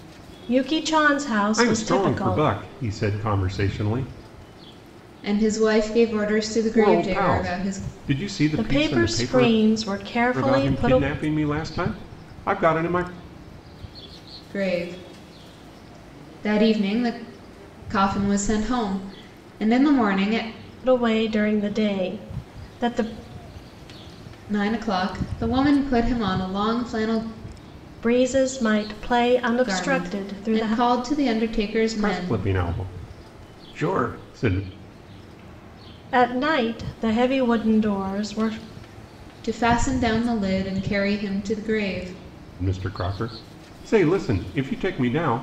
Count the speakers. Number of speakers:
3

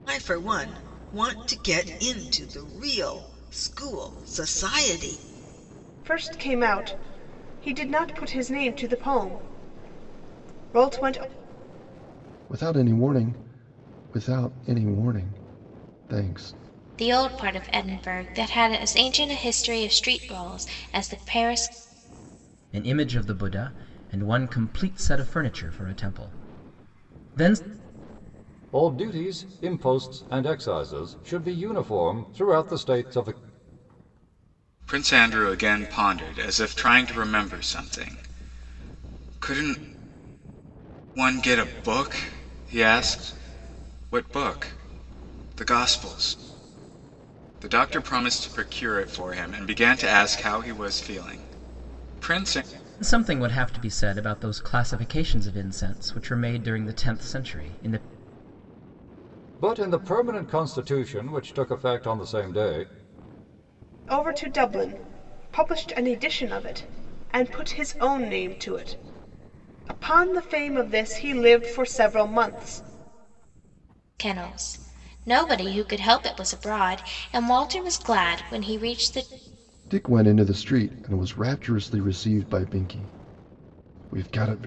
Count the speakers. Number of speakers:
7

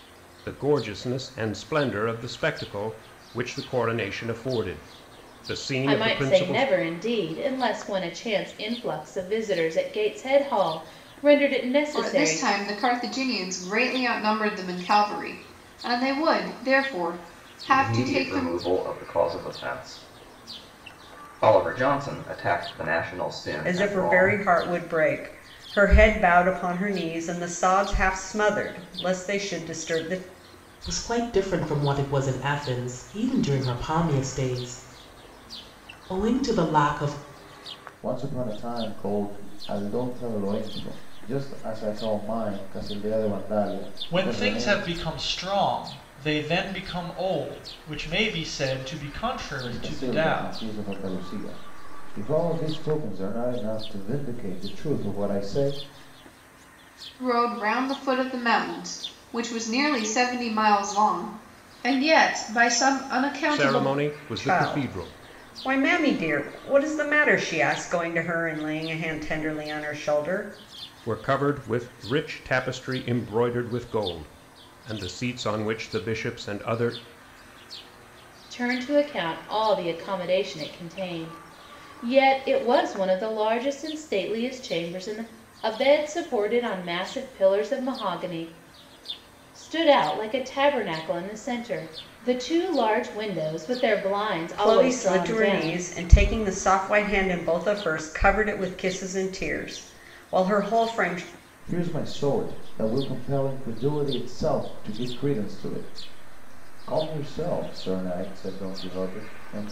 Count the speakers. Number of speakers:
8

